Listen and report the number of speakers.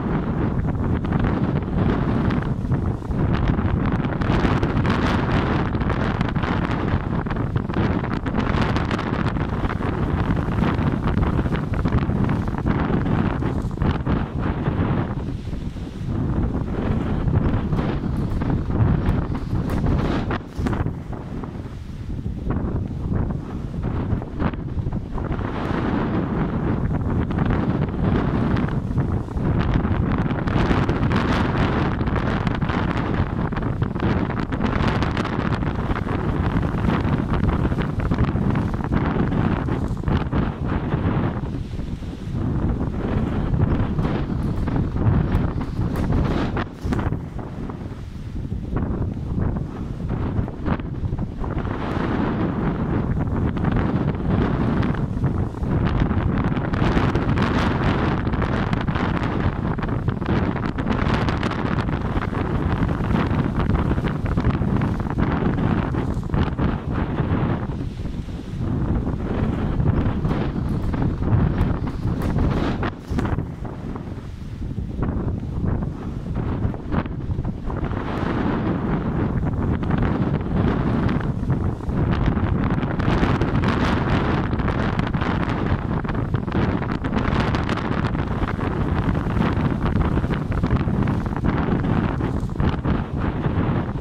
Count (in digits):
0